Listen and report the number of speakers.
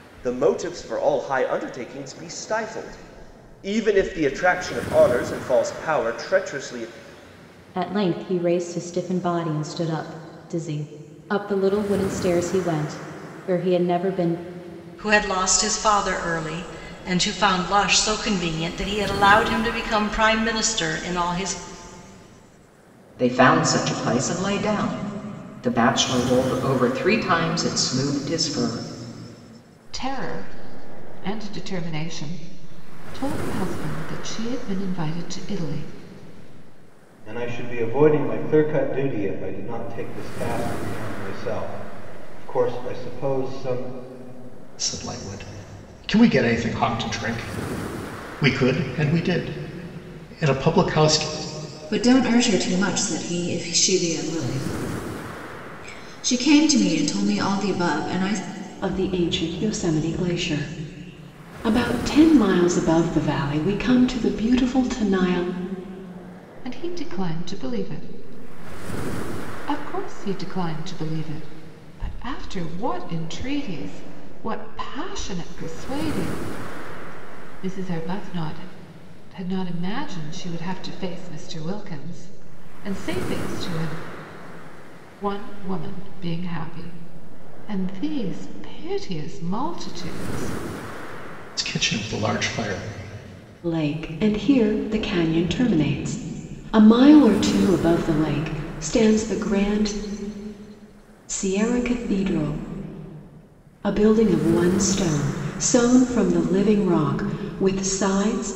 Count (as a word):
nine